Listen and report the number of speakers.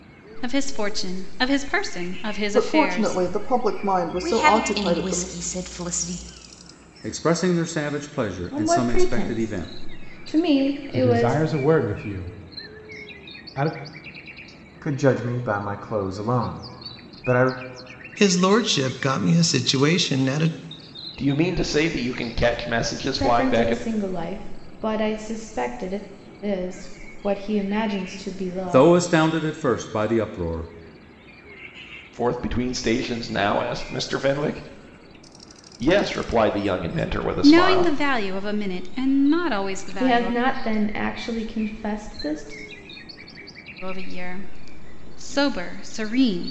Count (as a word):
nine